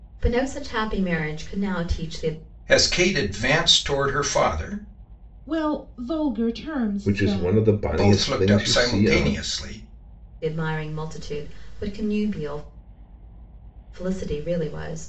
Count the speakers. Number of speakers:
4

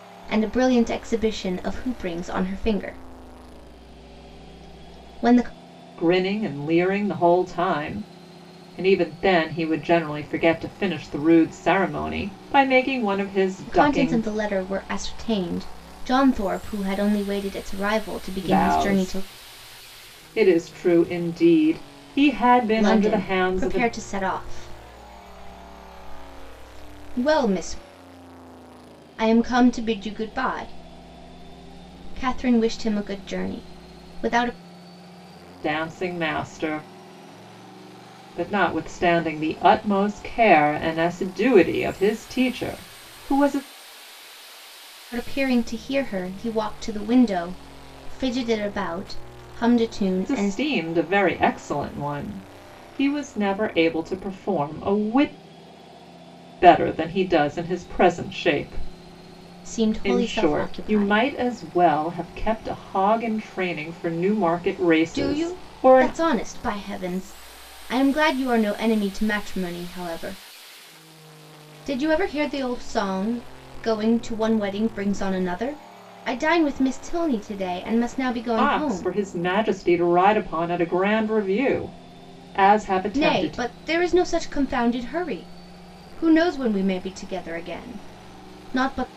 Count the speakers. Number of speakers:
2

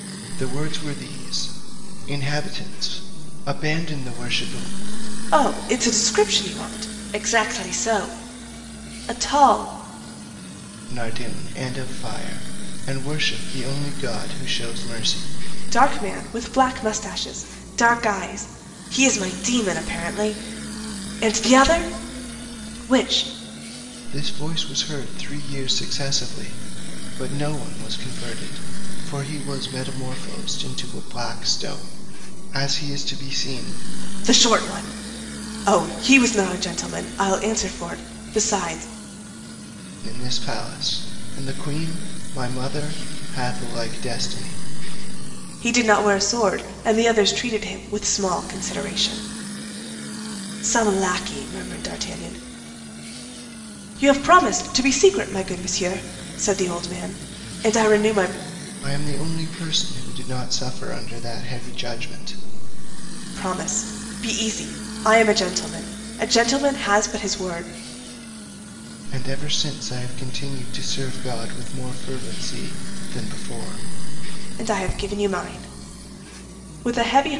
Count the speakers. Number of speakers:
2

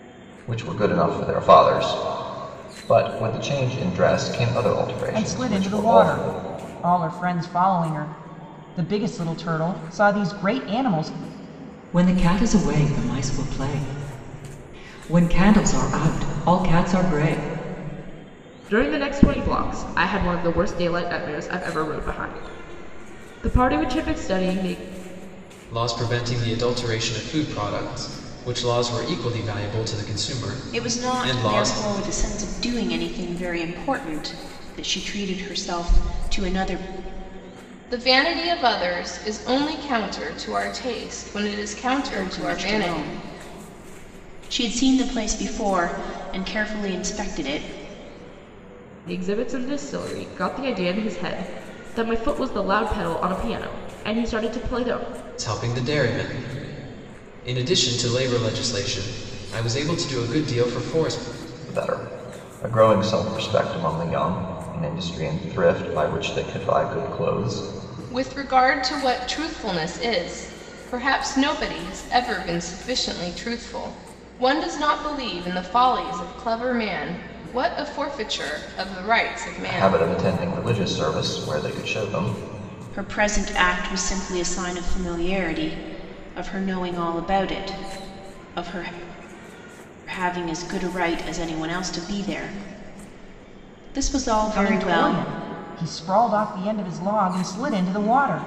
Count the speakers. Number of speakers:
7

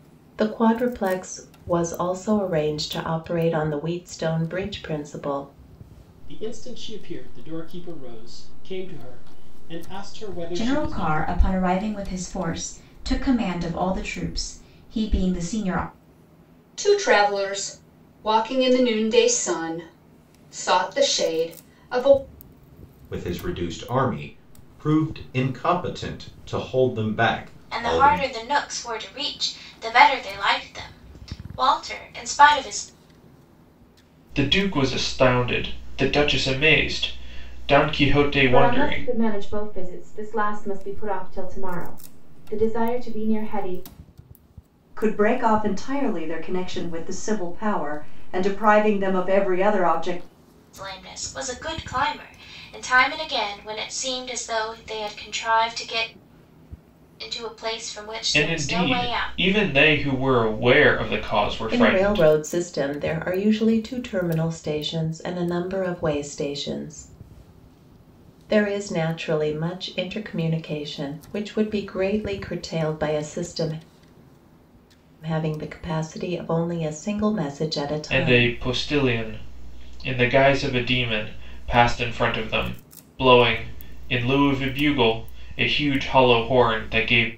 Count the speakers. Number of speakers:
9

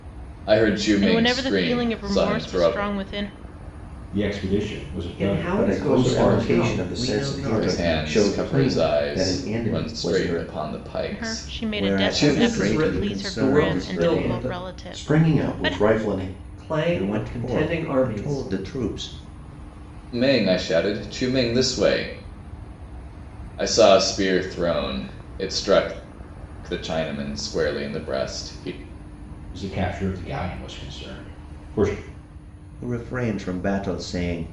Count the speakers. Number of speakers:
6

